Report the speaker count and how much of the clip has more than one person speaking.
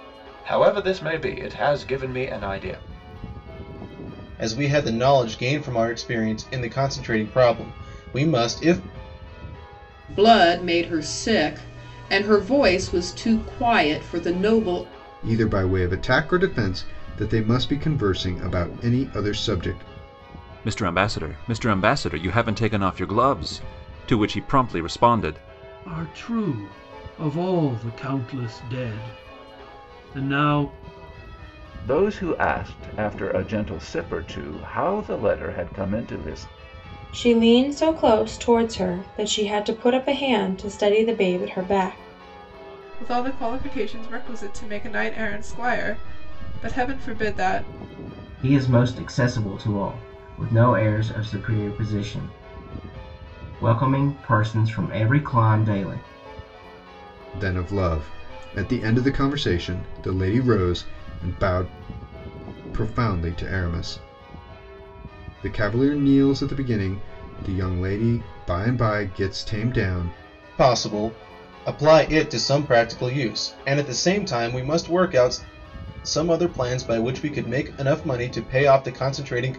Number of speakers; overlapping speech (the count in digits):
10, no overlap